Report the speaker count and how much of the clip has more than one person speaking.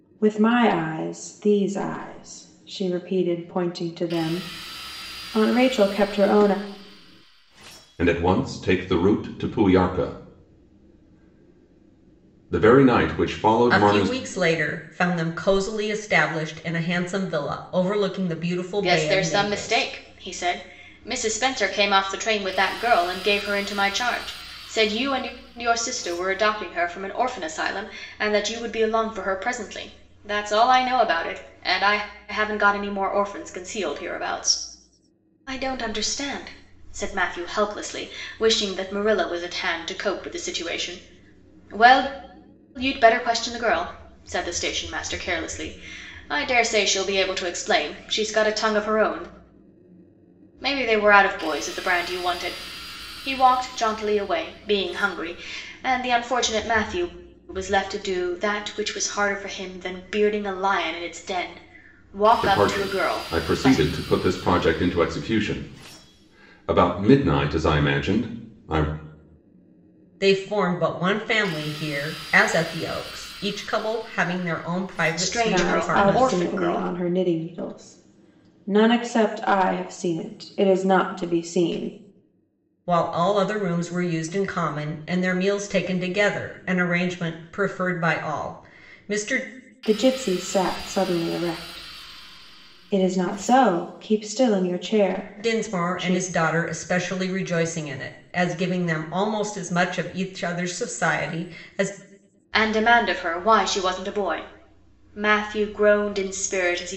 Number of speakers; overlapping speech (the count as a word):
four, about 5%